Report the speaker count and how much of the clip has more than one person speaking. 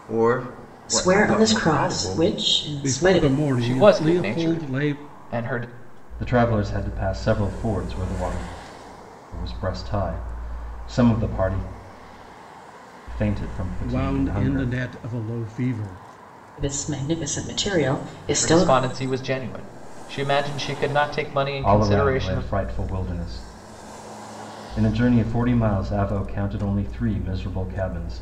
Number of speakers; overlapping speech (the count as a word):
five, about 19%